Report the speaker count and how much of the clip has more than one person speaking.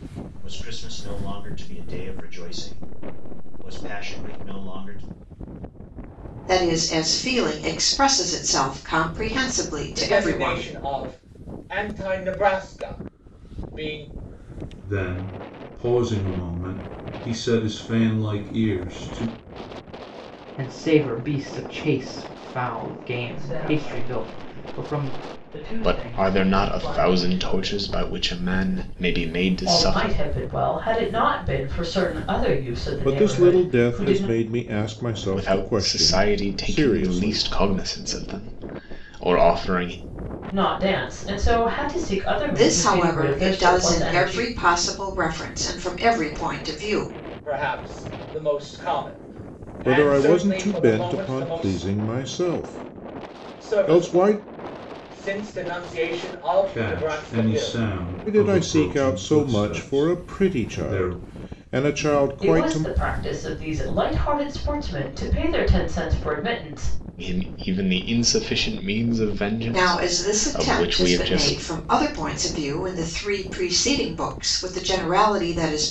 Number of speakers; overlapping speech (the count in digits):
9, about 27%